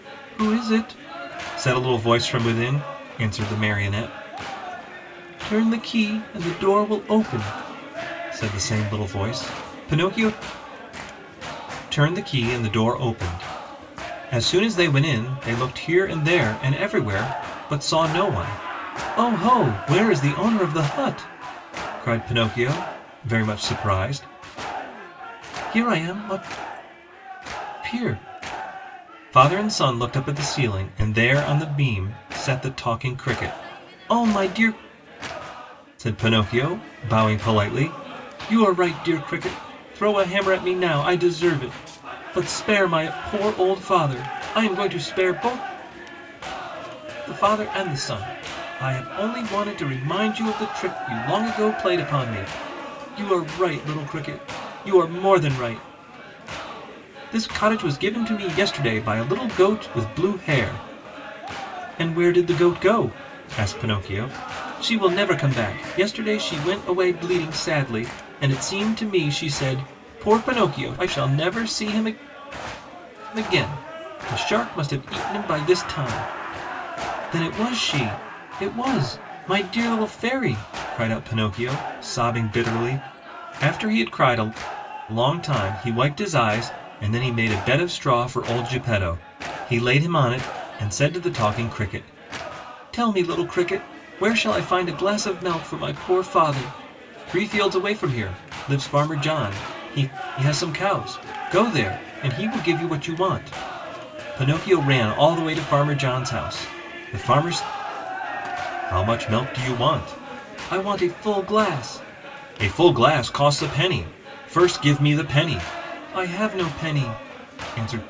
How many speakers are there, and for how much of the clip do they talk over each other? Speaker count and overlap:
1, no overlap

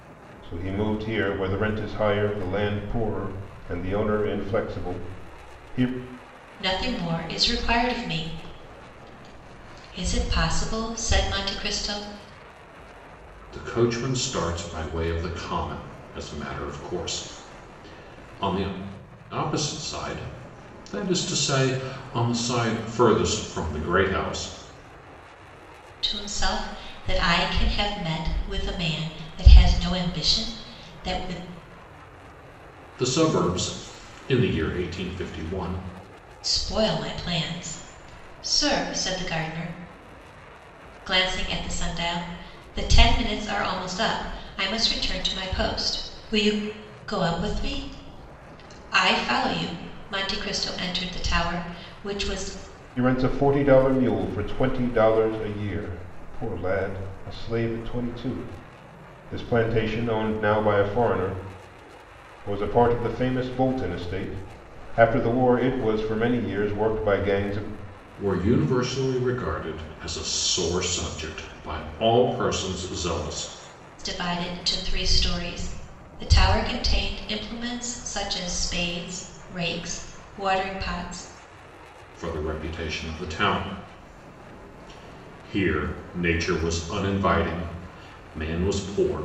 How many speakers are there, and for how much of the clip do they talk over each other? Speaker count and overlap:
3, no overlap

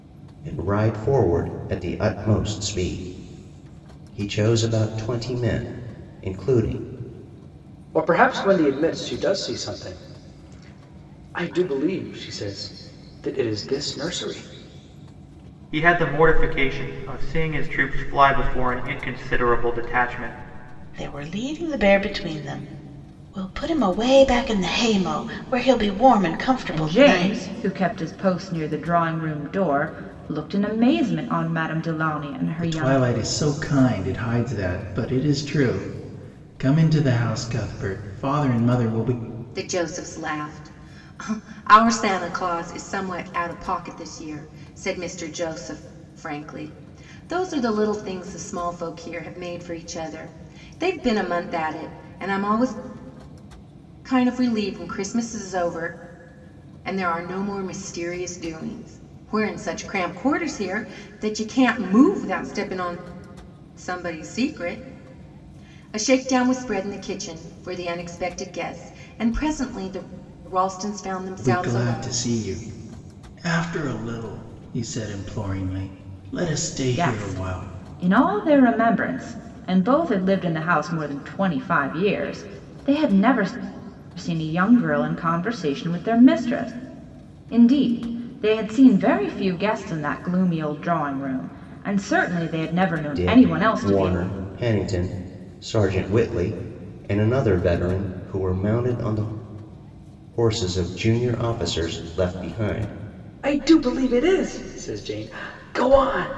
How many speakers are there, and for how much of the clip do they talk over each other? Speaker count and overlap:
7, about 4%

